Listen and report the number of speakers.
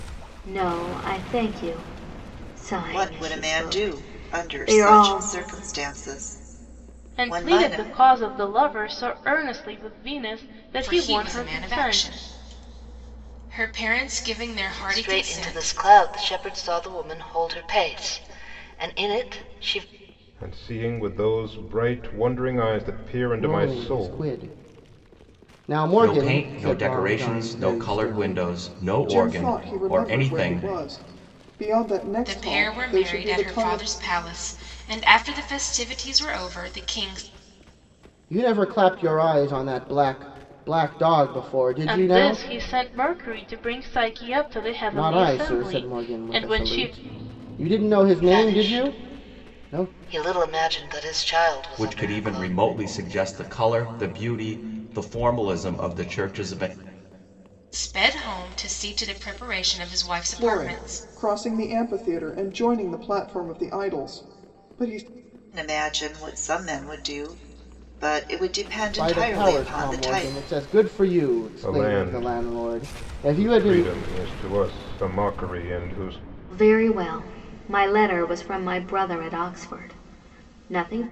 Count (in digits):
9